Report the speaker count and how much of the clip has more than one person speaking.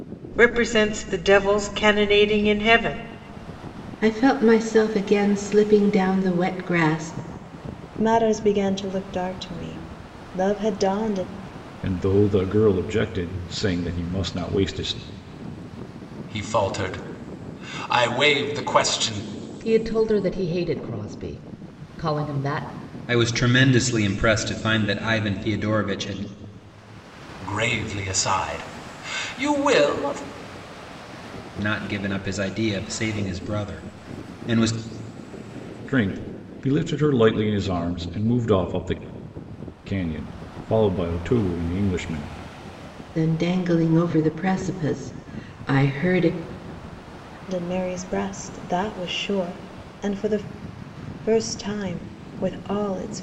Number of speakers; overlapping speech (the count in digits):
7, no overlap